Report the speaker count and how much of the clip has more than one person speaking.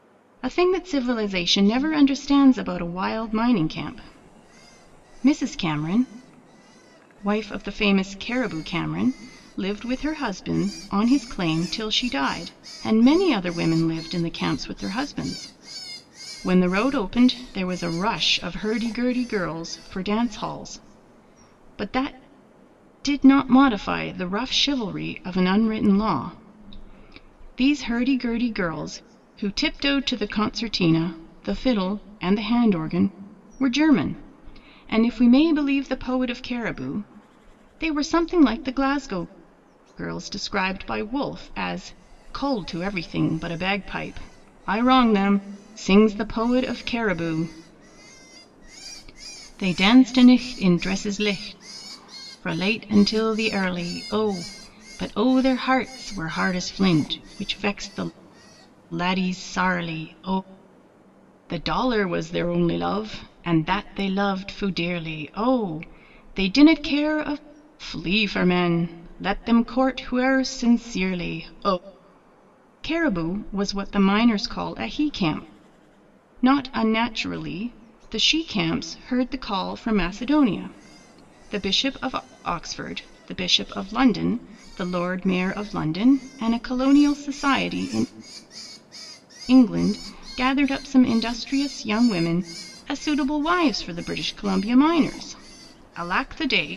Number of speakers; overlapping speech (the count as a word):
one, no overlap